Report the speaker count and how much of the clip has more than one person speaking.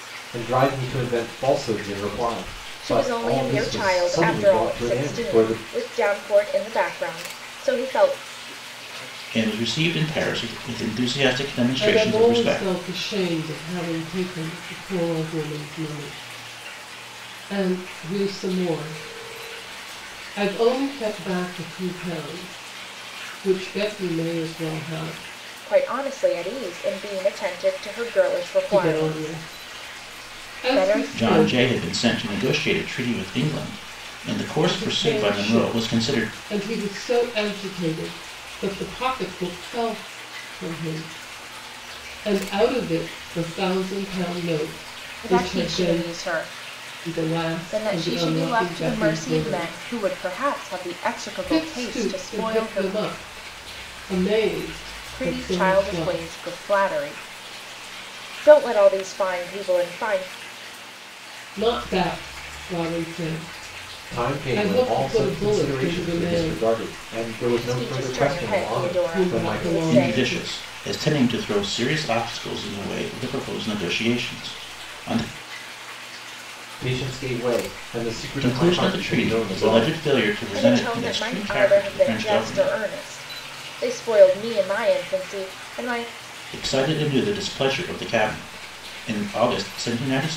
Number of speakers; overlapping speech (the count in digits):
4, about 27%